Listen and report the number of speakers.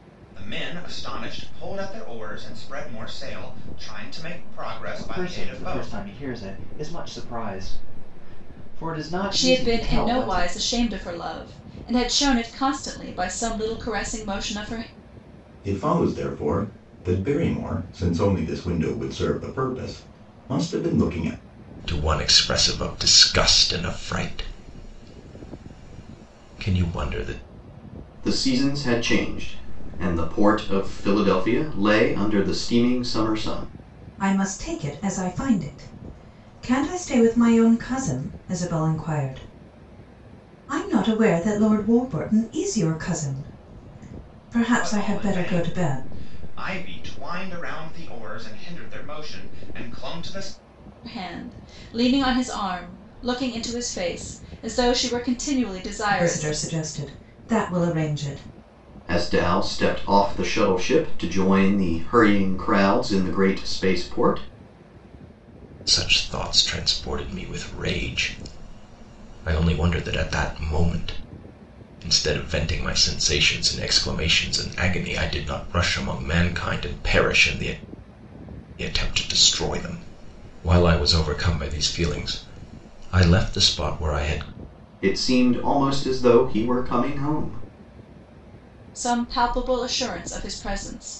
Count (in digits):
7